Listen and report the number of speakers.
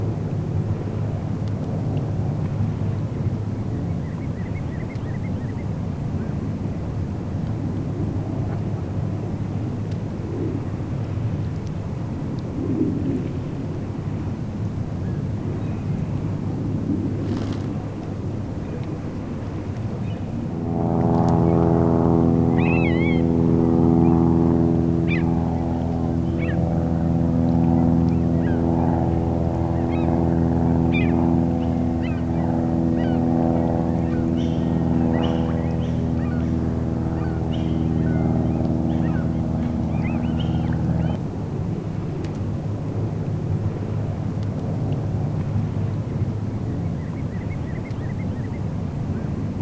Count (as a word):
zero